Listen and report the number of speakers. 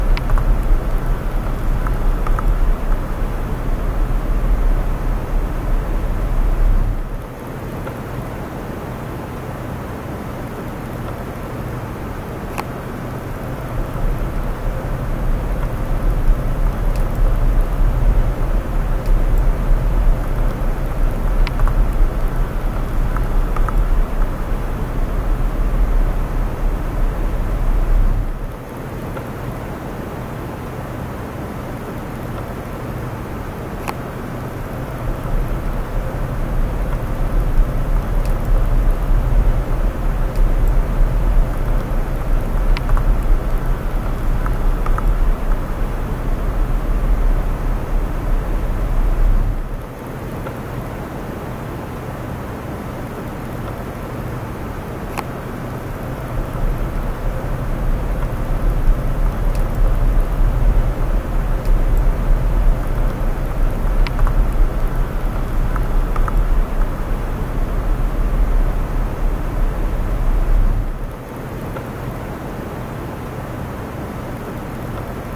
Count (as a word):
zero